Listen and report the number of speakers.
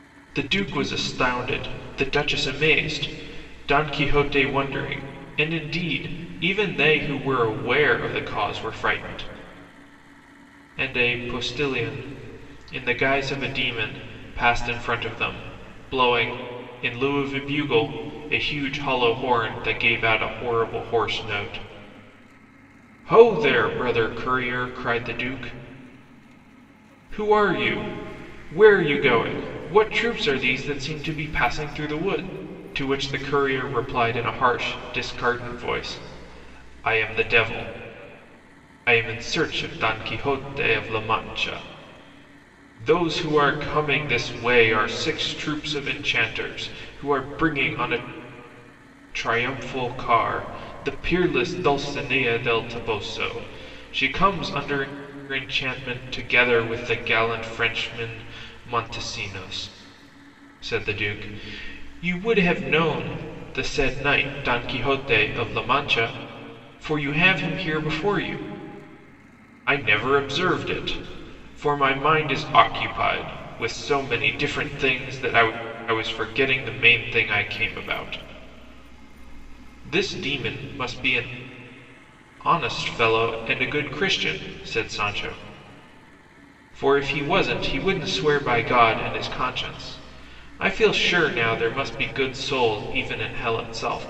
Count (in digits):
1